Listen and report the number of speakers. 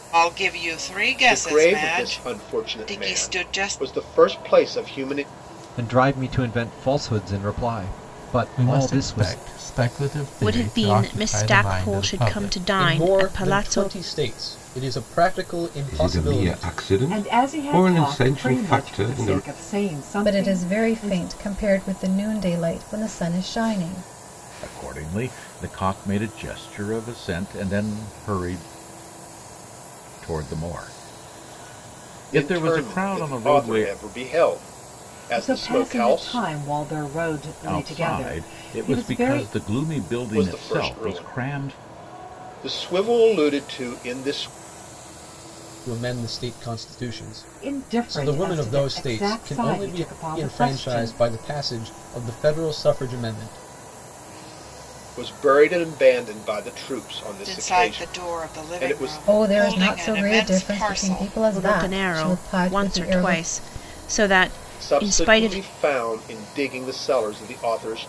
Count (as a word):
ten